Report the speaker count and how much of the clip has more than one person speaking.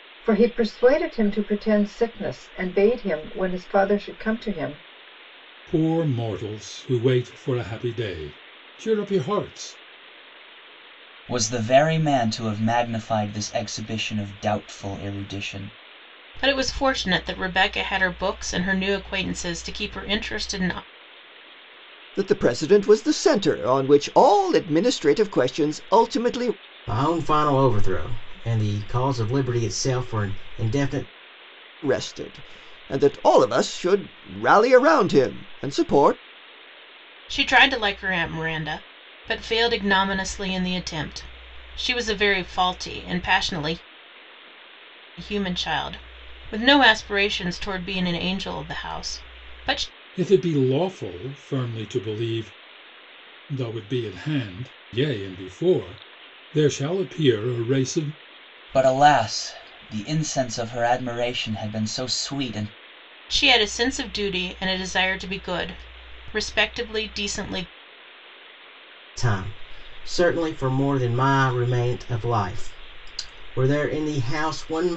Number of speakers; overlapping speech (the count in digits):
6, no overlap